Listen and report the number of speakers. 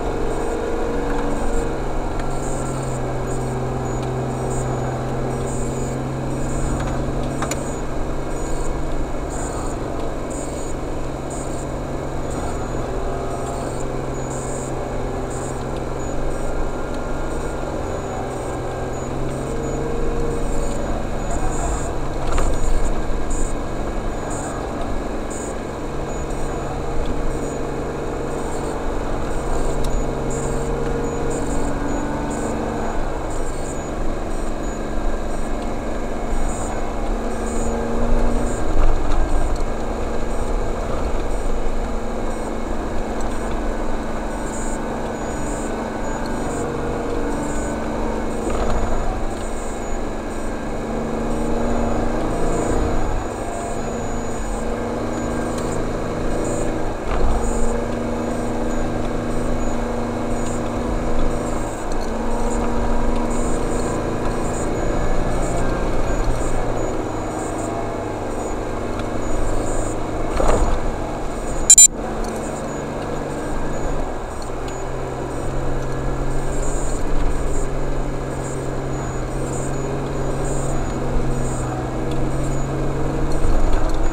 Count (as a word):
zero